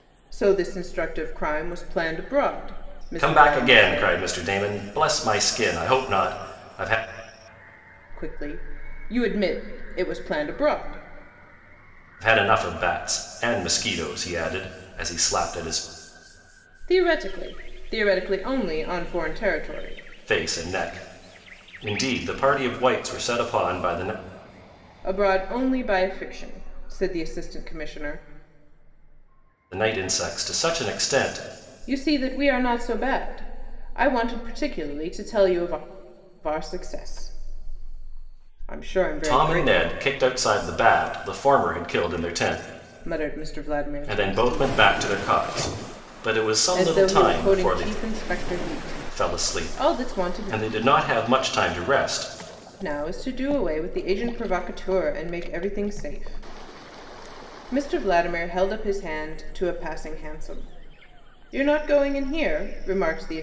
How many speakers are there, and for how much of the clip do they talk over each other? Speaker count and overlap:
2, about 9%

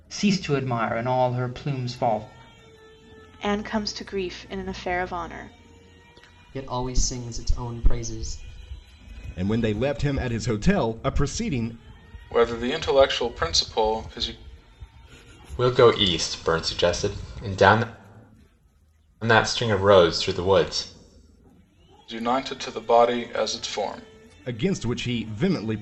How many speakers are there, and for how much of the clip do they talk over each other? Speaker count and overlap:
6, no overlap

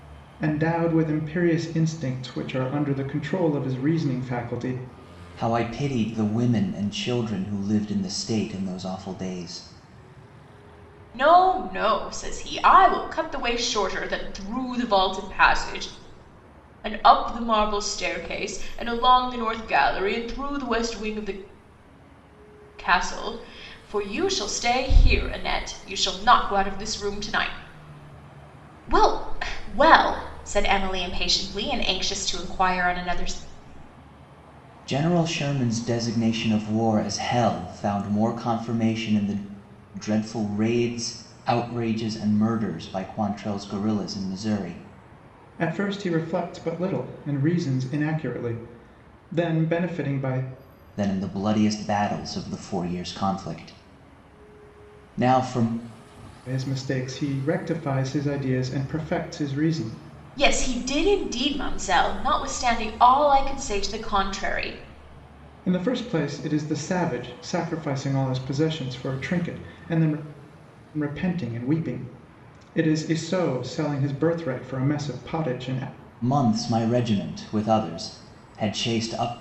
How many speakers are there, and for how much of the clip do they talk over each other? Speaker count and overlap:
3, no overlap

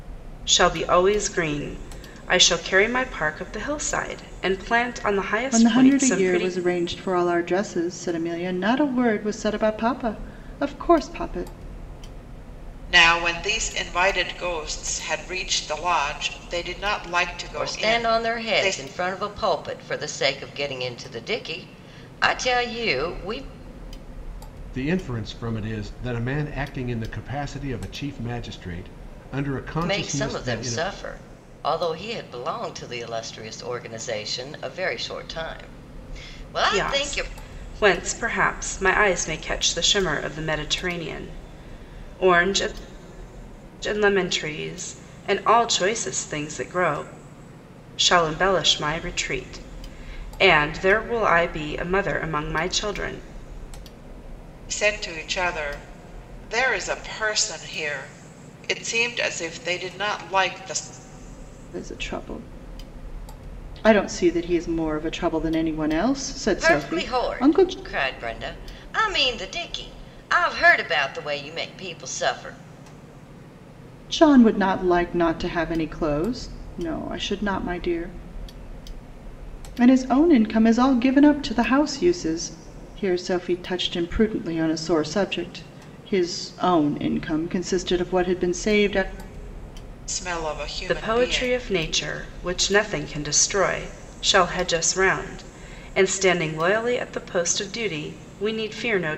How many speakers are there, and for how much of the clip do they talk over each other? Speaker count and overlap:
5, about 6%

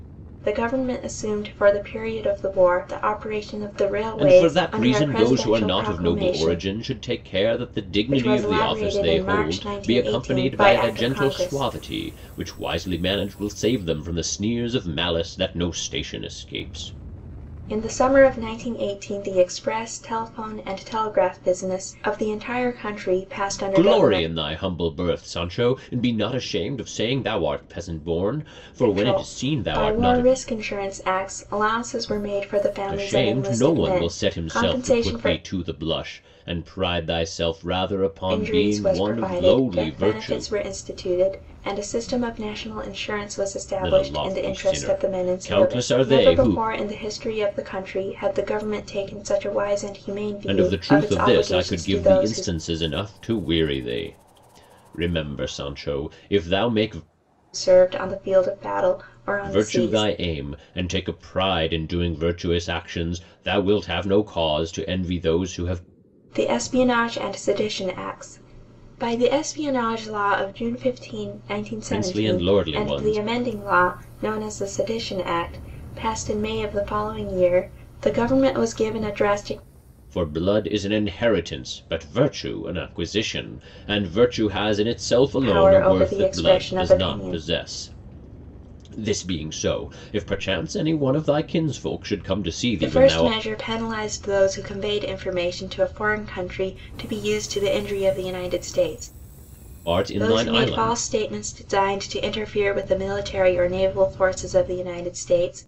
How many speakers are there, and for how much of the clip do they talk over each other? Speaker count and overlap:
2, about 23%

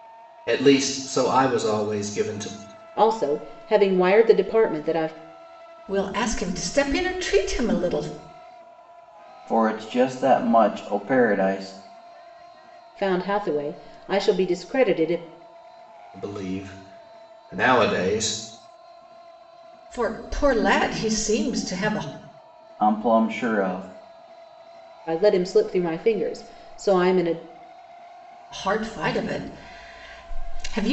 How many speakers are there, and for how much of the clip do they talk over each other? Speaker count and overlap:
4, no overlap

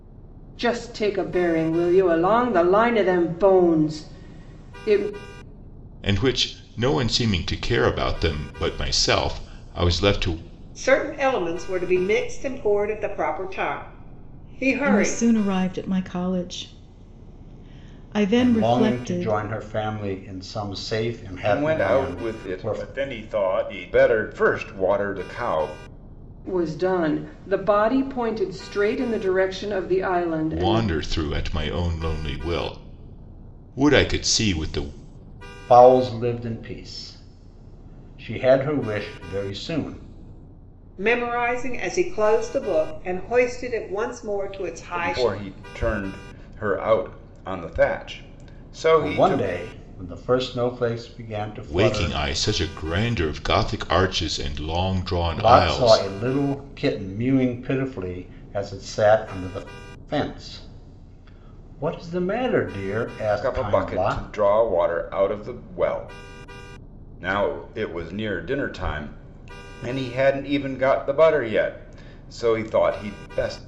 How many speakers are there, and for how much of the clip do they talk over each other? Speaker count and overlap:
6, about 9%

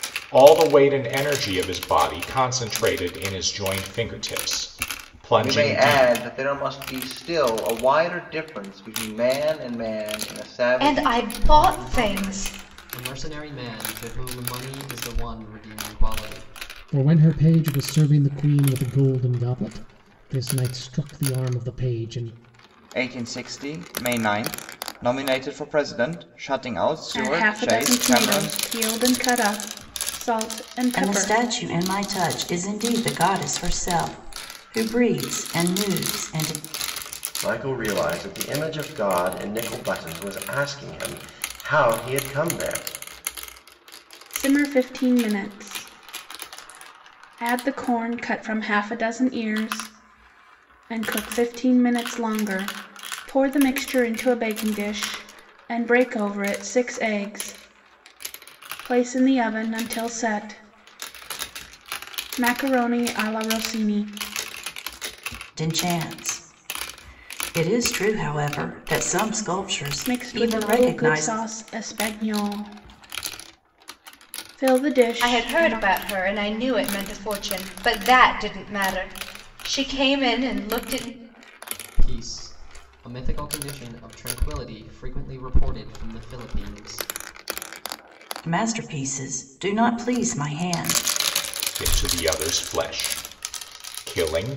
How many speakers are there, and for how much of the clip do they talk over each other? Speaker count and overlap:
9, about 7%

